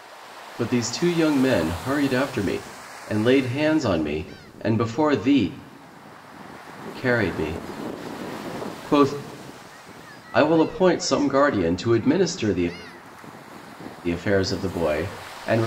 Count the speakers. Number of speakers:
1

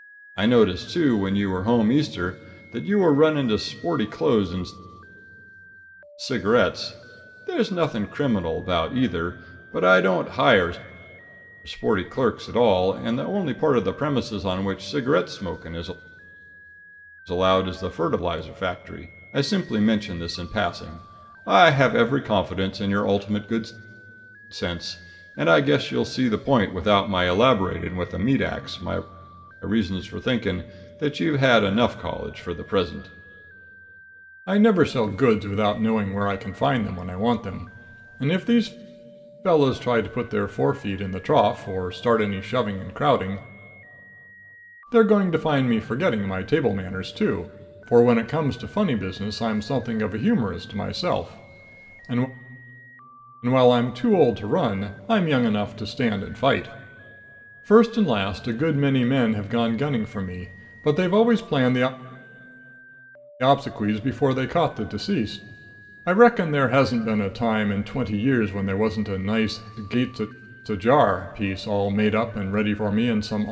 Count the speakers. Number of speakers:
1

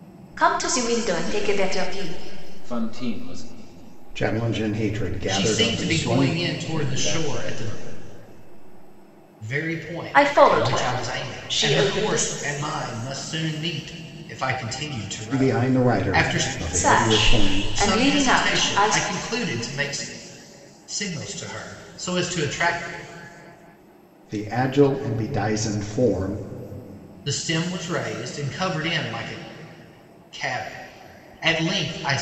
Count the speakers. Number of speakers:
4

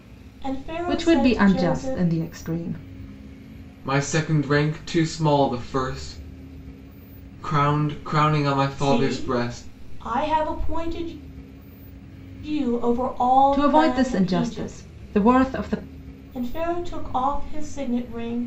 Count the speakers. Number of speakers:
3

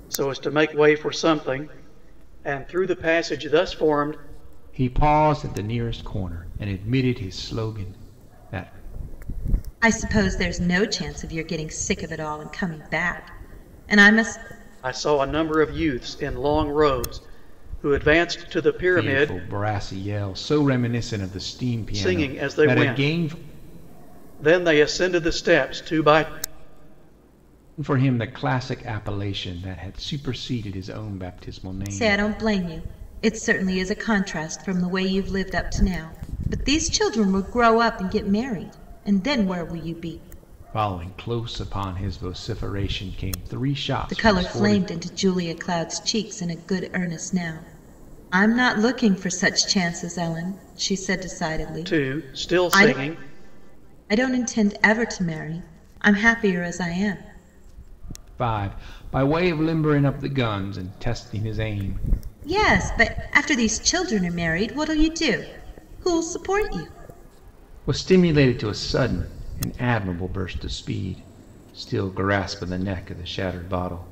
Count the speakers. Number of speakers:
3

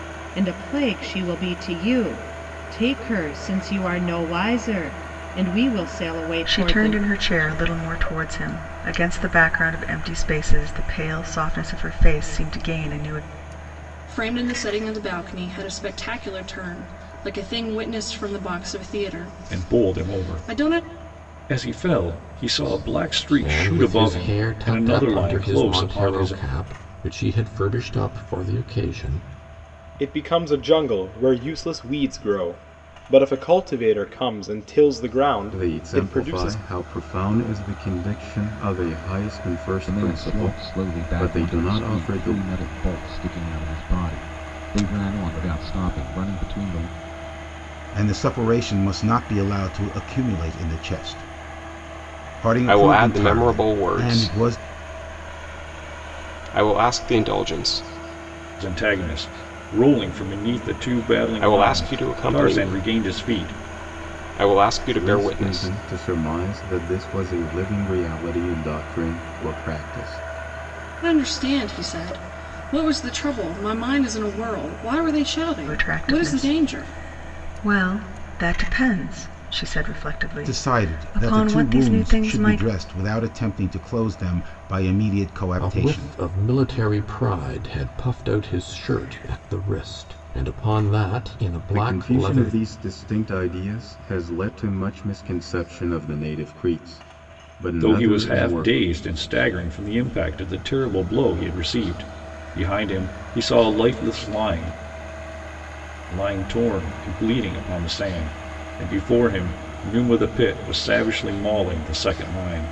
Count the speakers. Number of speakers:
10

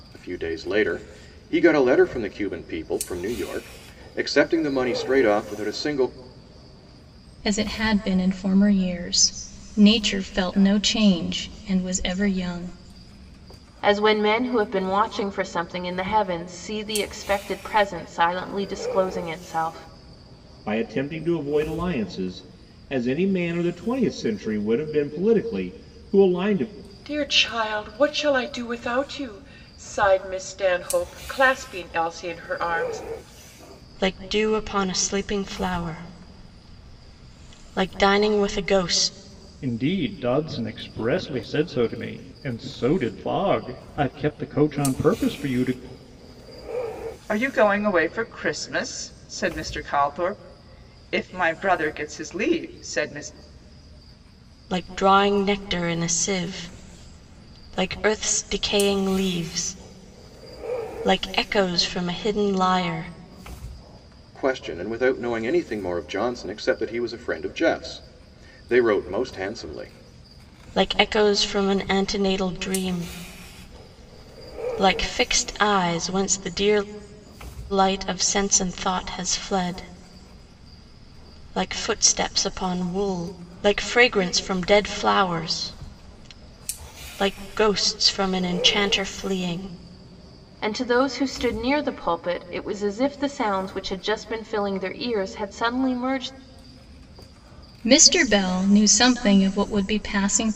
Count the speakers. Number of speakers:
8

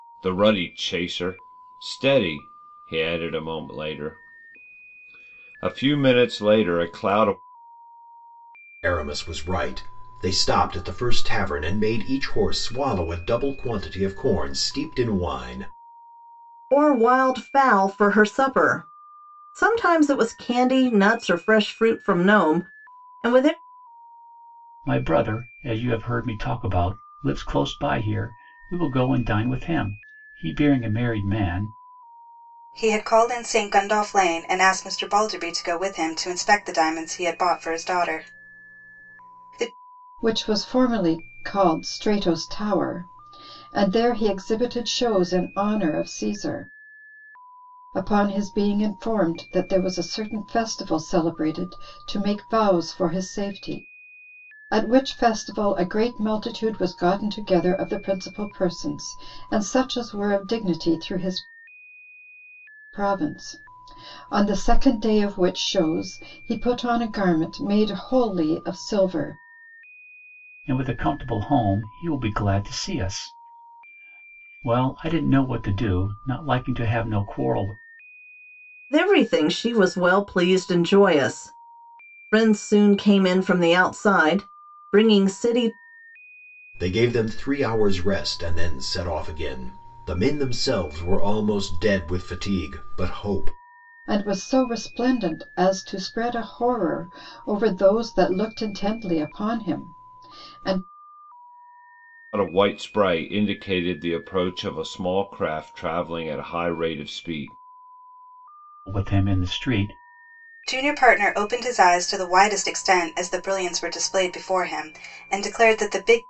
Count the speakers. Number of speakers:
6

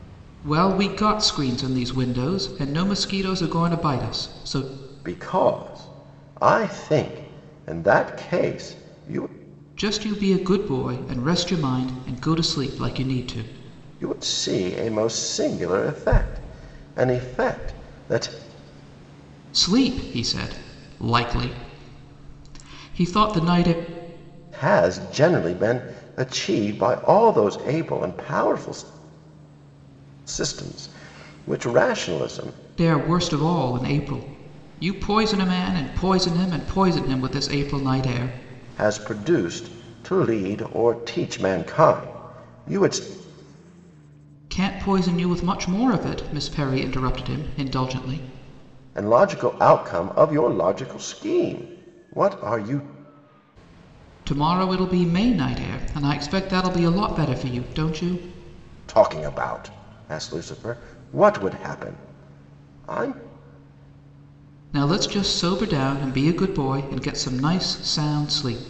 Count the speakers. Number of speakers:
2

